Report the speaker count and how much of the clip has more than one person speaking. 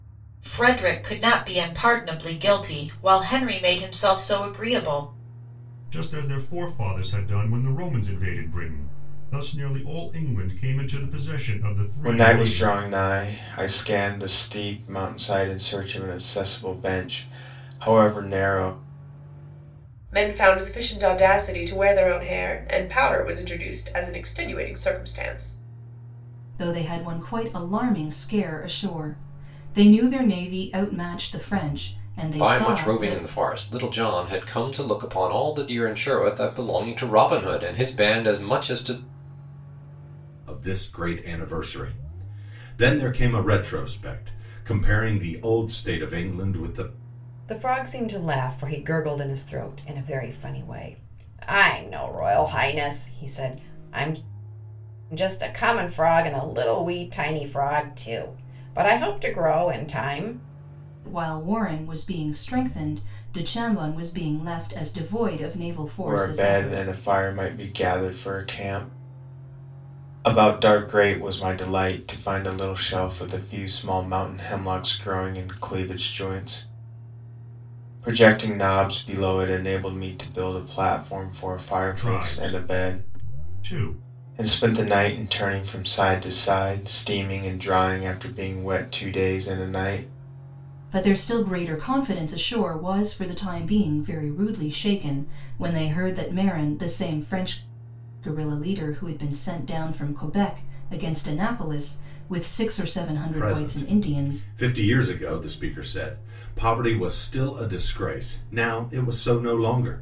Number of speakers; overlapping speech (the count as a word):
eight, about 4%